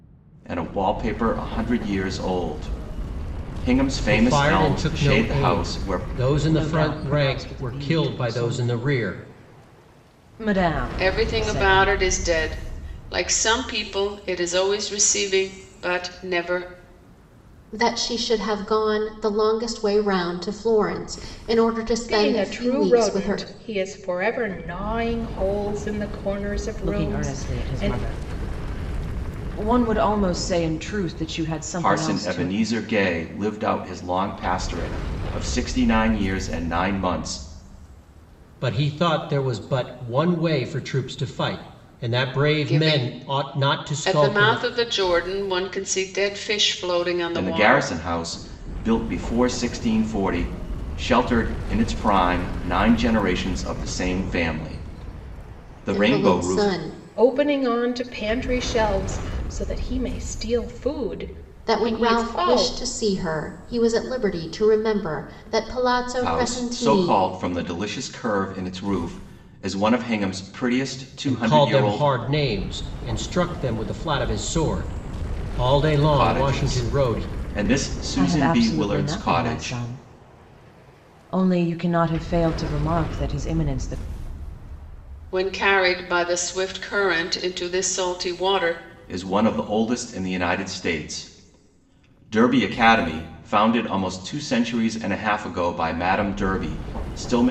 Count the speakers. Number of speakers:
six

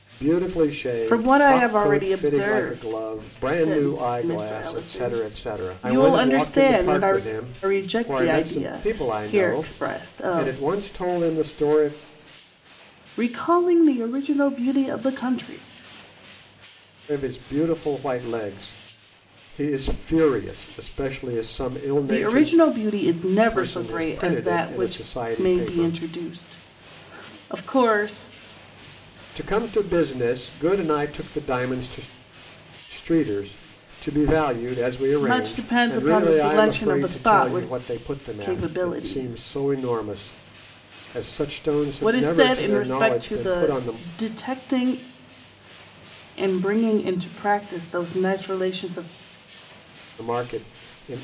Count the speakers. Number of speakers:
two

